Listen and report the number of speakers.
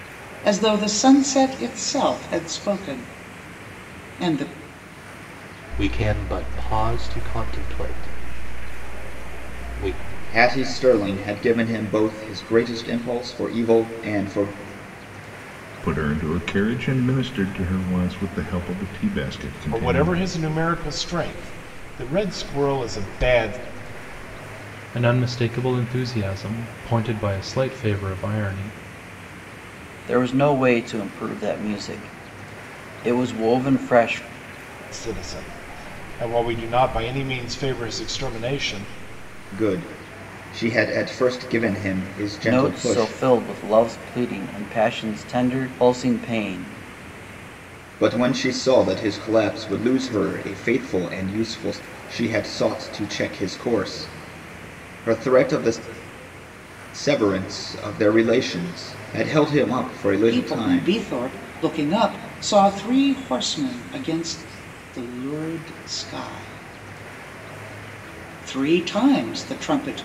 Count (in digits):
7